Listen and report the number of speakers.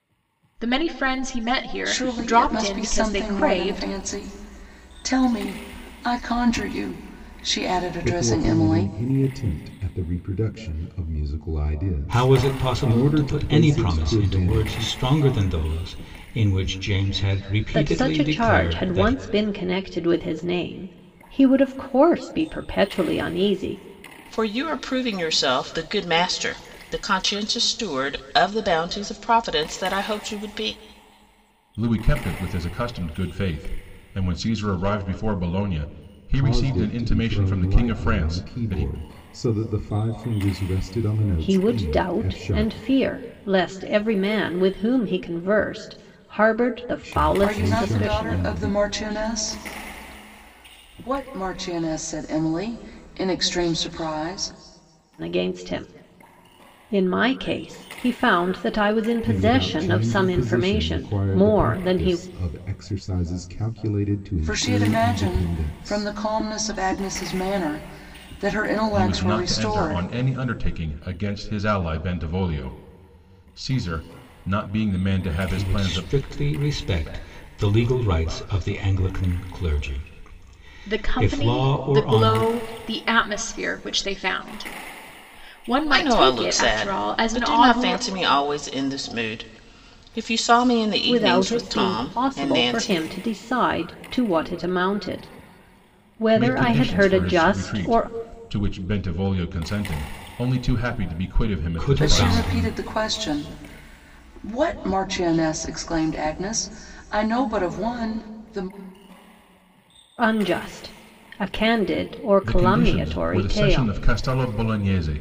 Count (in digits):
7